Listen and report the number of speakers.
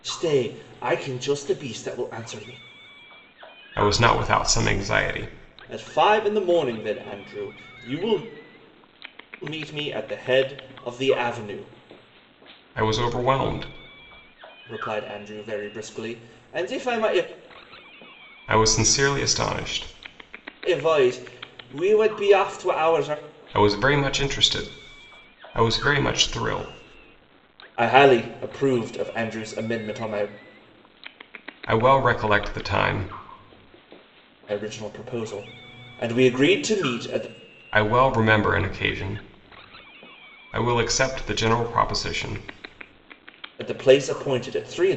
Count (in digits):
2